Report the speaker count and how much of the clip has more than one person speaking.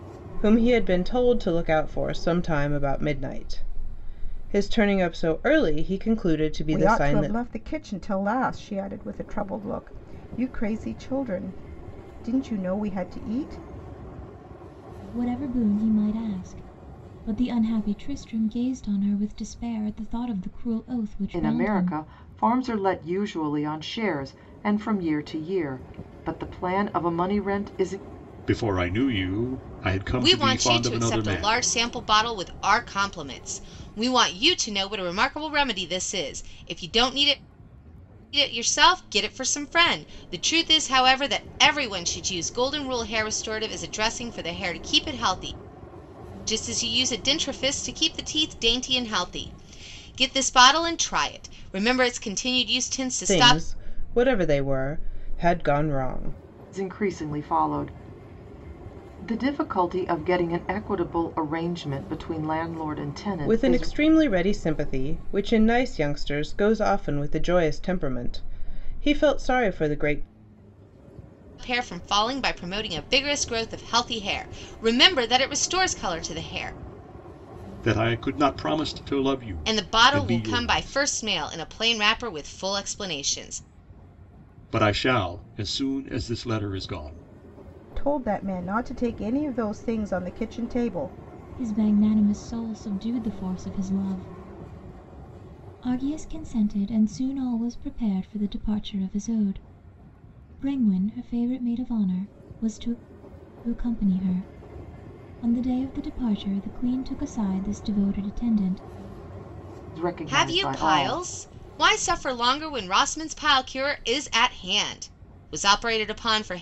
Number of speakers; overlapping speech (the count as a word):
six, about 5%